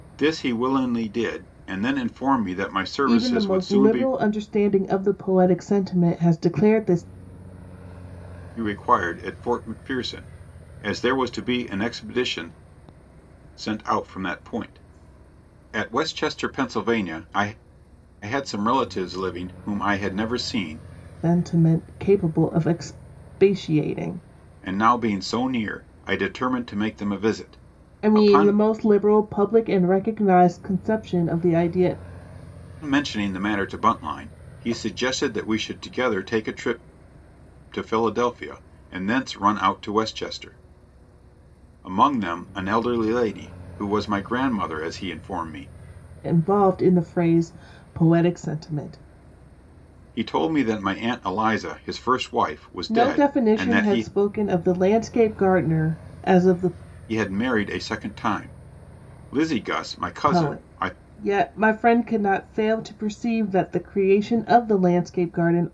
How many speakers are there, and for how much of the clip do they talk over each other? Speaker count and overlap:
2, about 5%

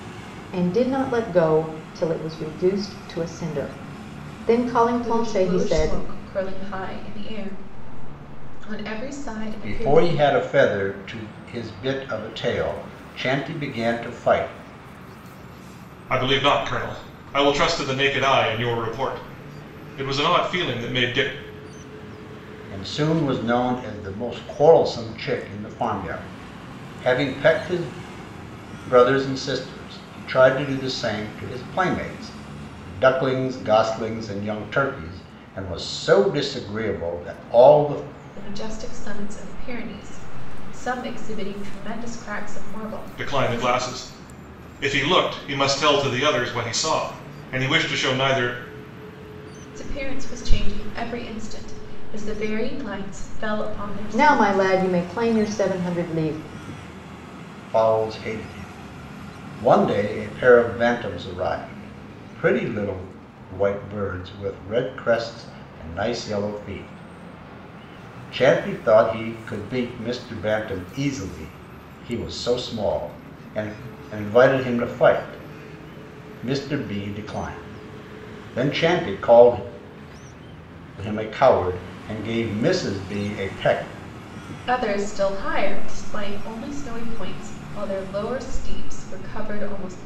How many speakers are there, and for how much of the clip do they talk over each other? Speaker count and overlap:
4, about 3%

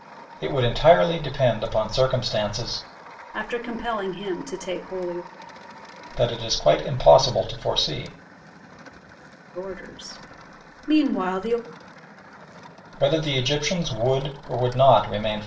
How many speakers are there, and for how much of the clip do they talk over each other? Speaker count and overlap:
2, no overlap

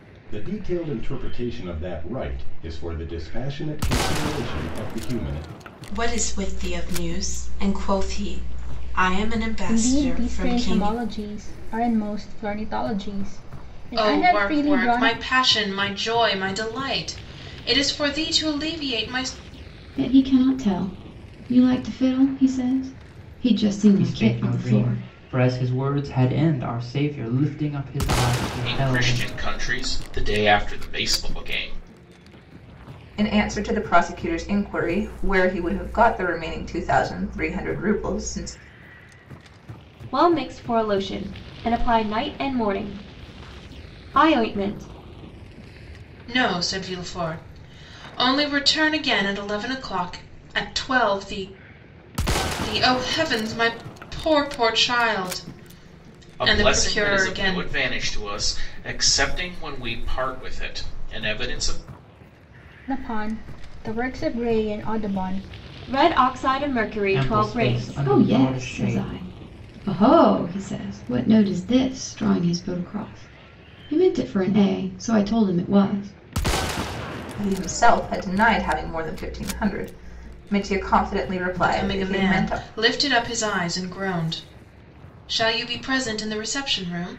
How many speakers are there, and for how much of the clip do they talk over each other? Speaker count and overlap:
9, about 10%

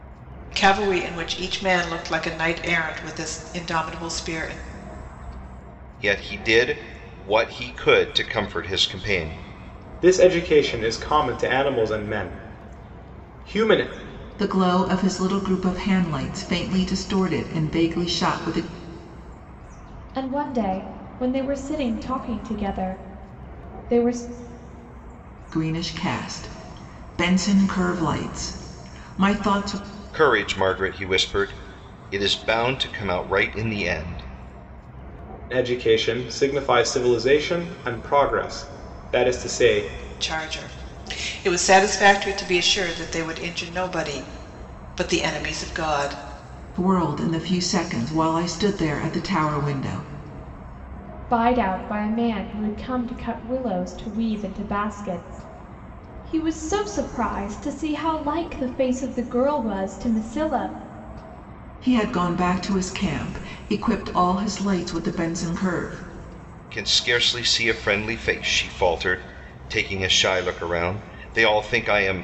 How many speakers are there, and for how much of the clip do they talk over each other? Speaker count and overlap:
5, no overlap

